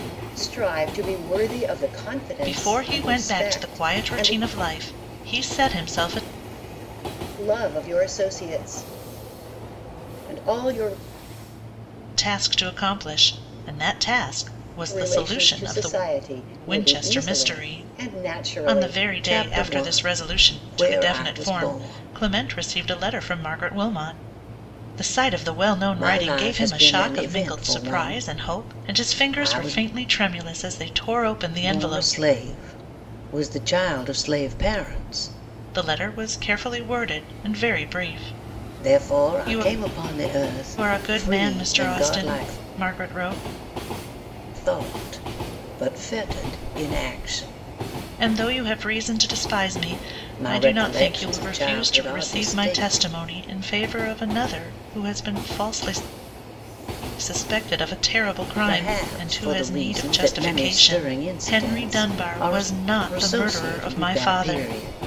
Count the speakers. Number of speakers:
2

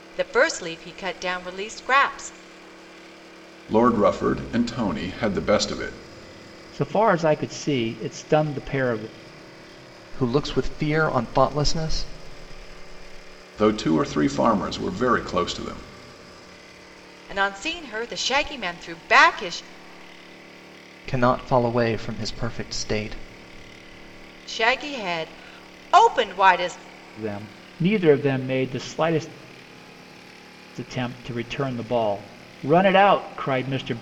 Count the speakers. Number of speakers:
4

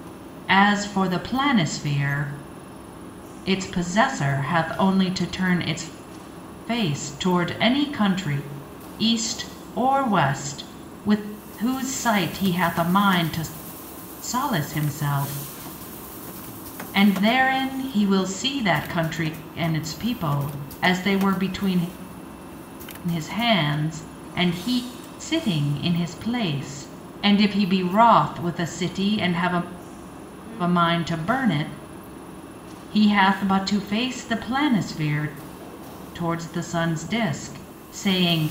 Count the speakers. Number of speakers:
1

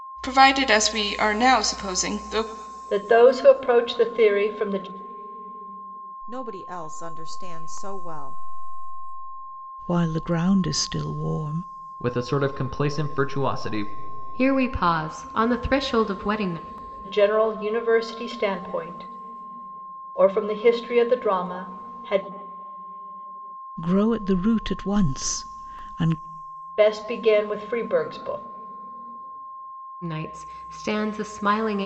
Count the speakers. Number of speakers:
6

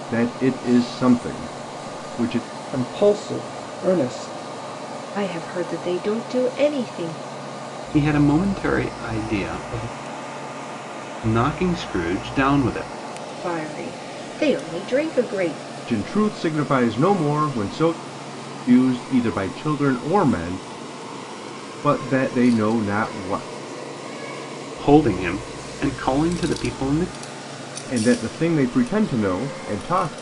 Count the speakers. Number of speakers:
4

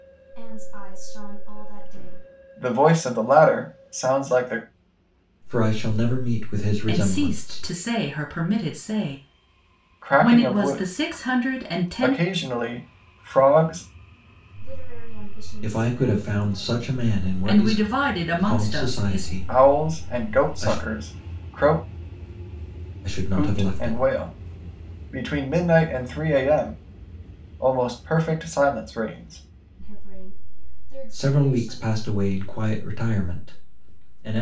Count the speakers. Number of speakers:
4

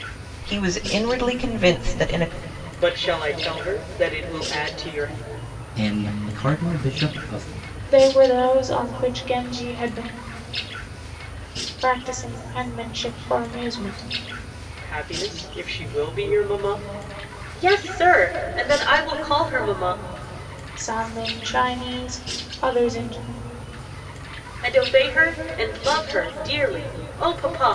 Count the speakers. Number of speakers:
4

